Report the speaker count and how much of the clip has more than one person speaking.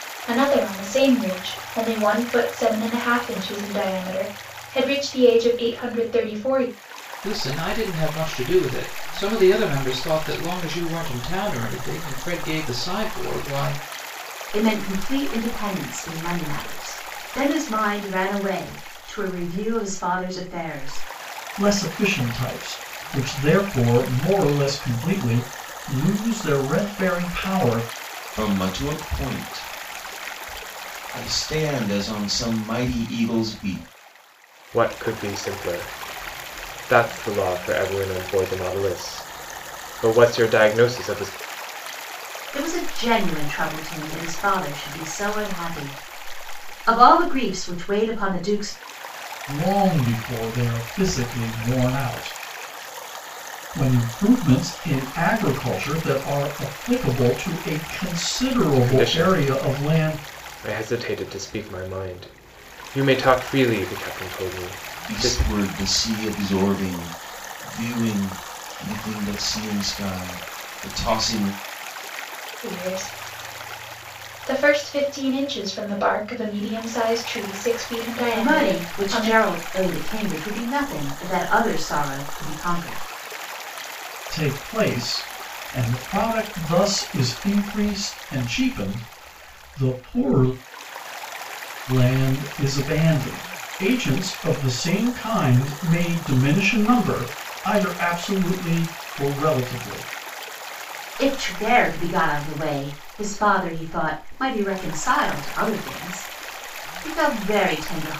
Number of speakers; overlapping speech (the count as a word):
six, about 3%